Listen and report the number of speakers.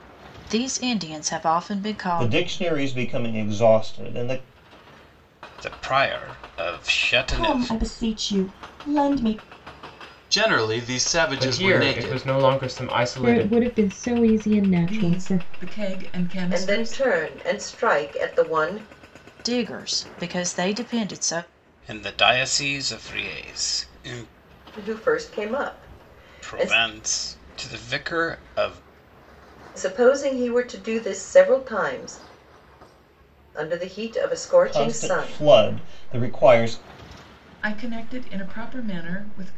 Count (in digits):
9